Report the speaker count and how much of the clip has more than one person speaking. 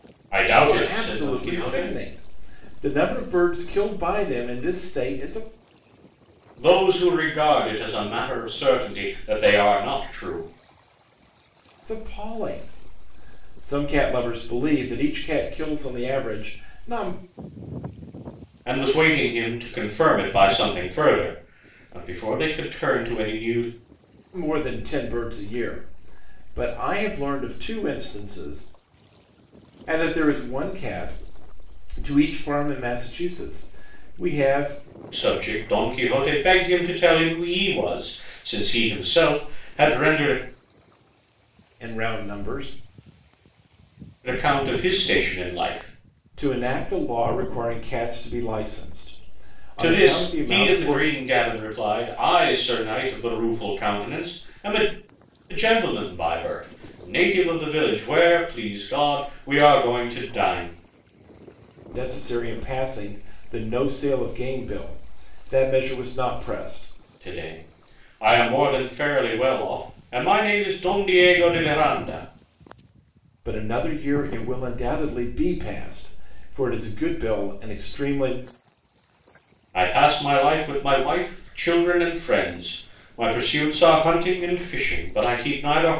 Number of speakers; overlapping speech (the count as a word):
two, about 3%